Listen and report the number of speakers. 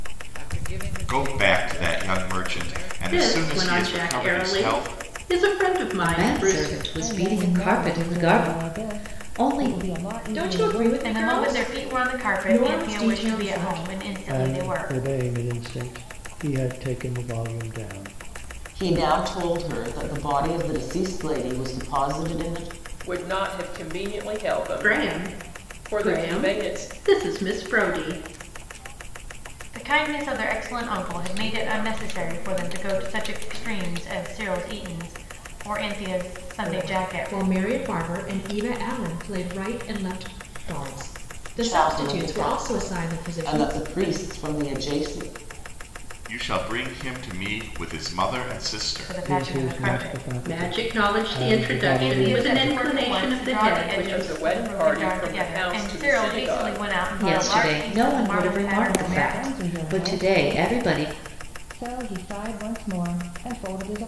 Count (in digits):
10